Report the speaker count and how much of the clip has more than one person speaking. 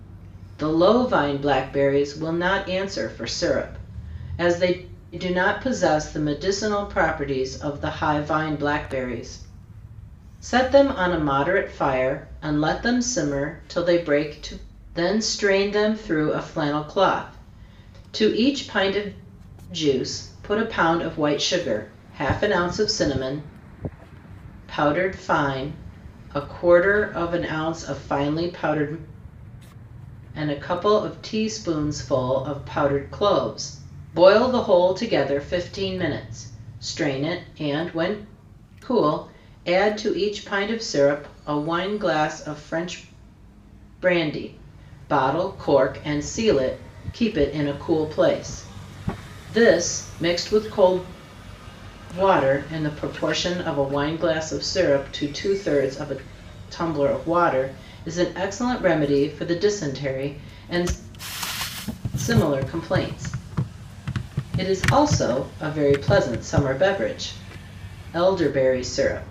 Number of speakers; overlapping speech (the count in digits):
1, no overlap